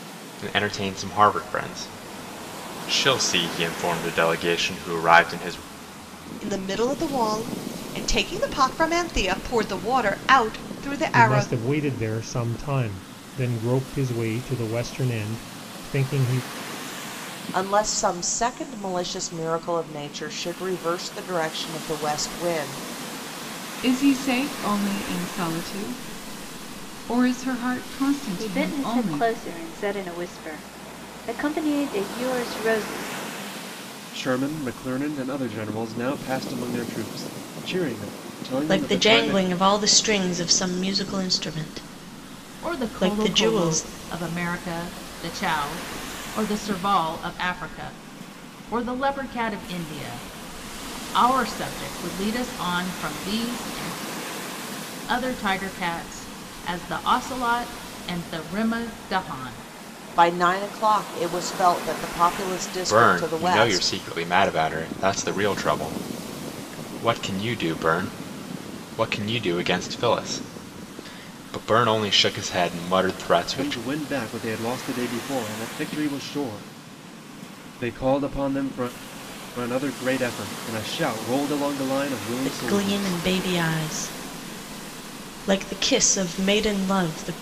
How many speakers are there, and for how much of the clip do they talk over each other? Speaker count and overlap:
9, about 7%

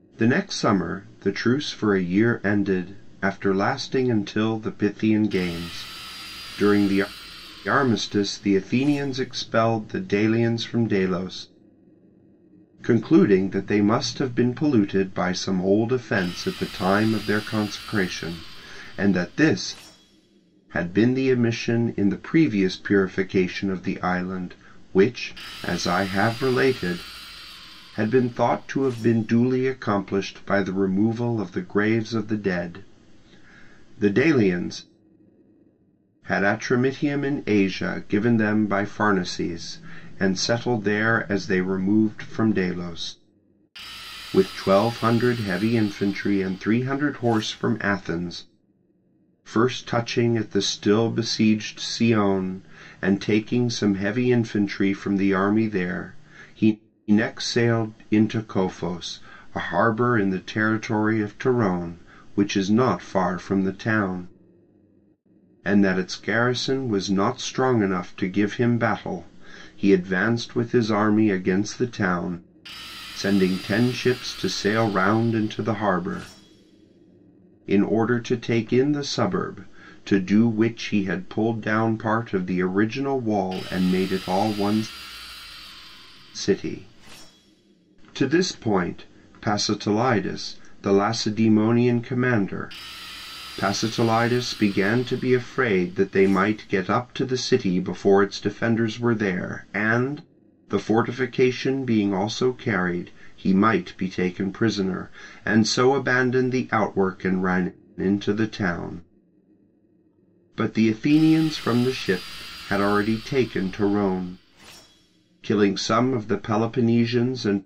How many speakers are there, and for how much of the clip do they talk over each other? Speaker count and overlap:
1, no overlap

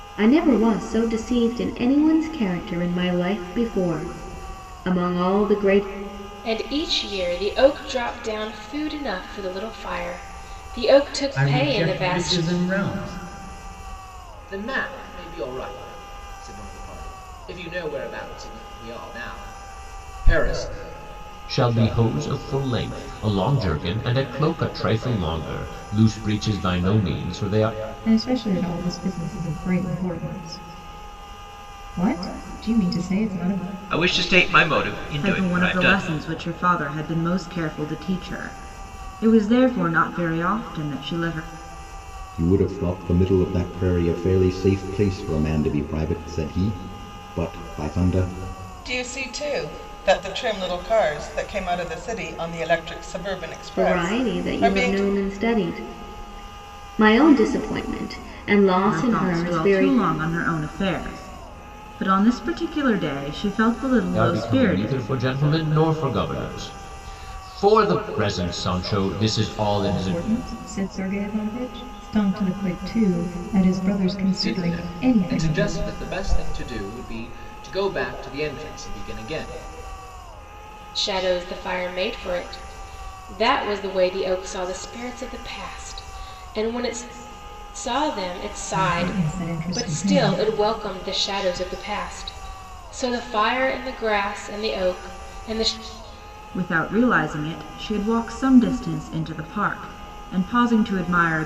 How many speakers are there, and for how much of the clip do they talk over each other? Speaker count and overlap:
10, about 8%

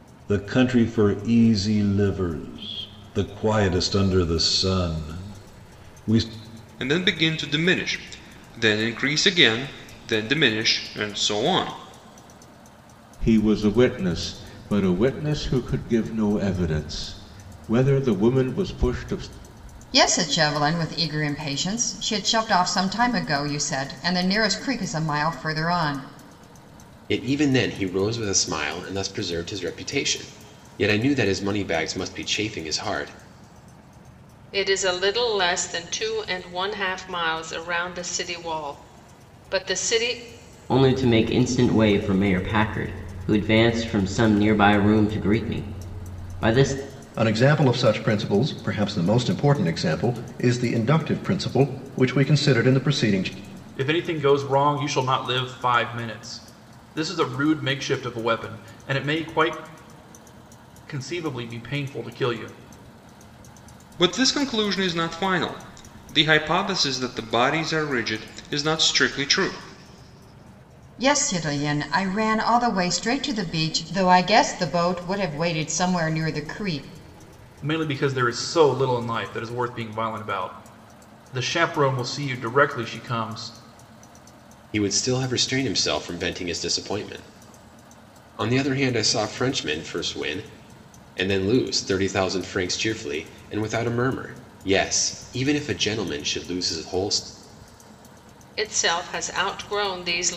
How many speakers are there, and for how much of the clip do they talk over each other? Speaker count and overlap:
9, no overlap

